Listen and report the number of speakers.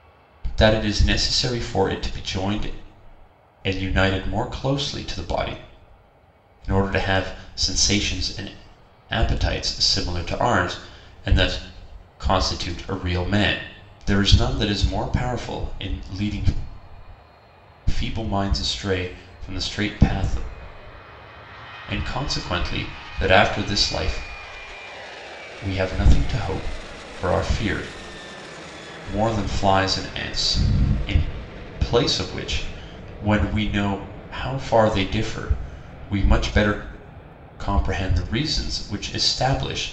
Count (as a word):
one